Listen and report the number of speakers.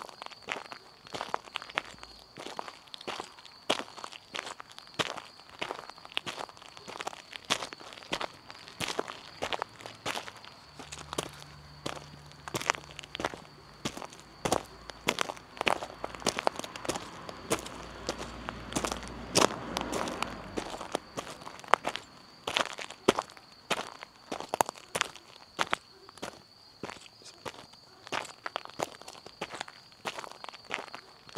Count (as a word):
zero